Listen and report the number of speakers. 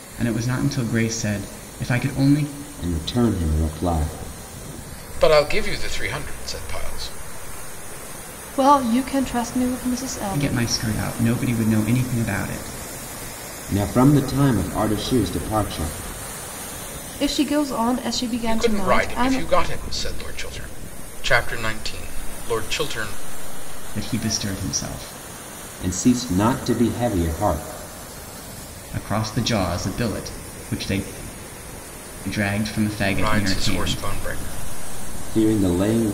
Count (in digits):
4